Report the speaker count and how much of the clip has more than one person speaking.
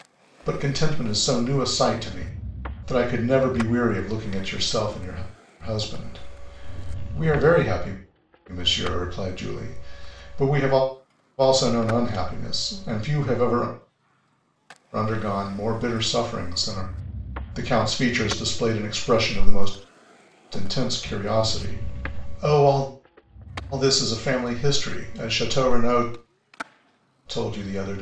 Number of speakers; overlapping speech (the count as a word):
one, no overlap